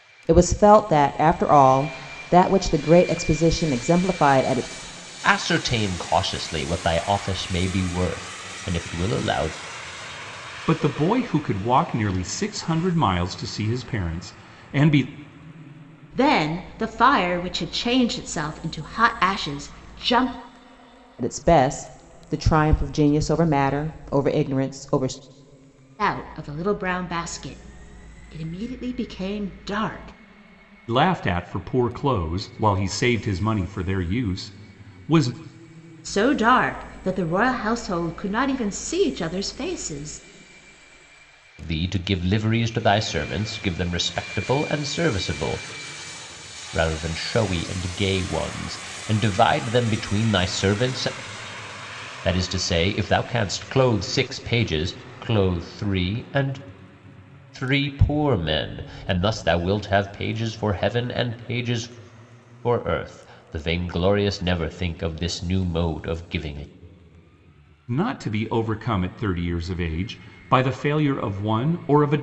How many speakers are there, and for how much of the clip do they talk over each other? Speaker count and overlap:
4, no overlap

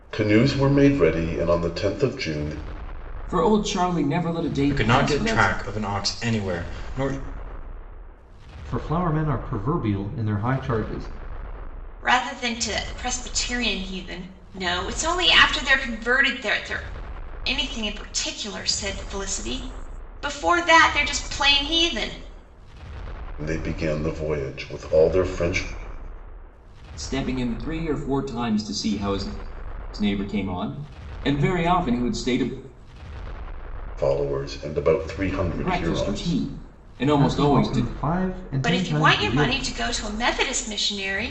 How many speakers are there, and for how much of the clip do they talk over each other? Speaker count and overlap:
5, about 8%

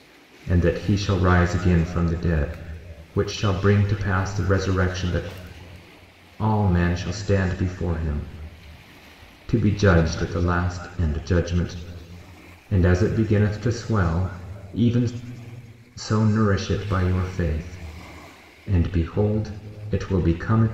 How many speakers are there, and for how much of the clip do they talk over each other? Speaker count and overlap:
1, no overlap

